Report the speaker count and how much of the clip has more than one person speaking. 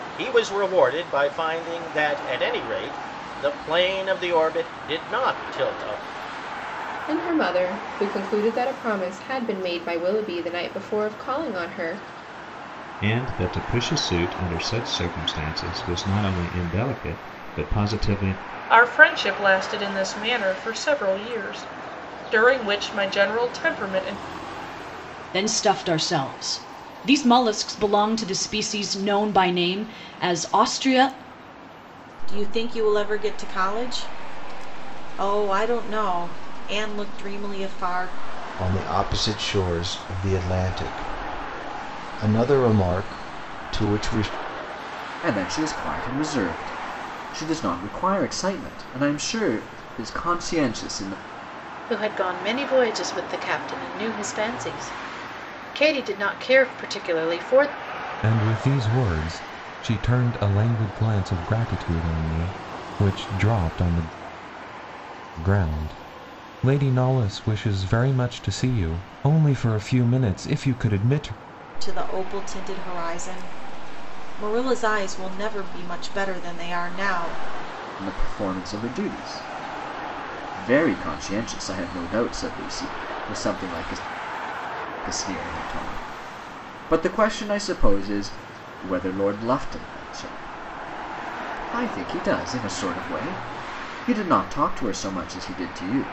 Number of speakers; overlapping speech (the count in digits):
10, no overlap